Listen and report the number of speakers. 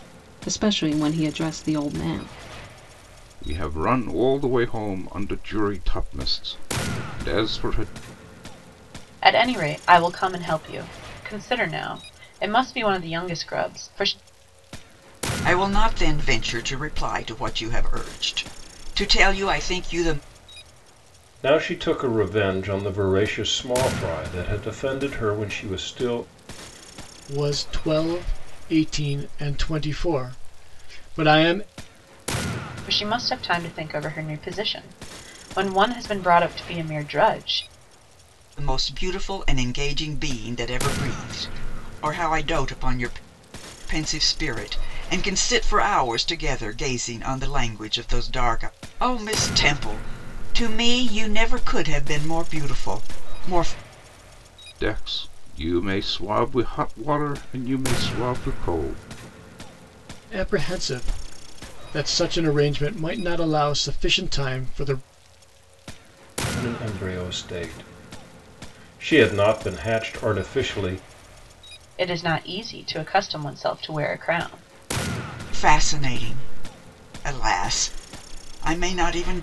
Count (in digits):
6